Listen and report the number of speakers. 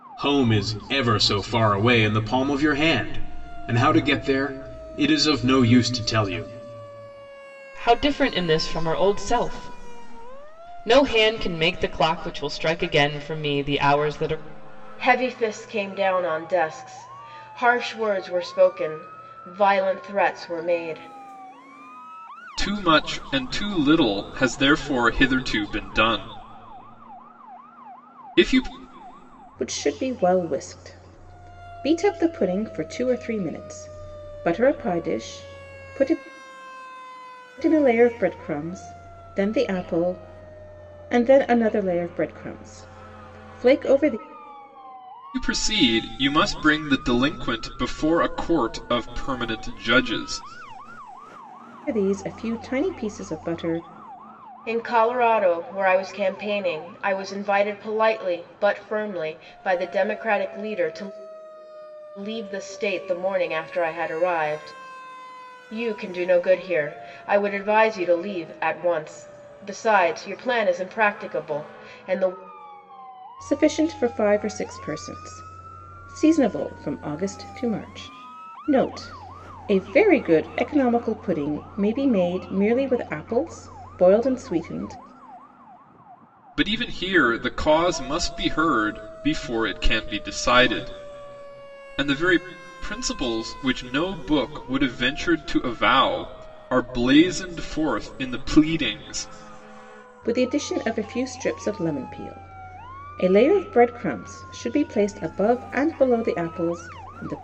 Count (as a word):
five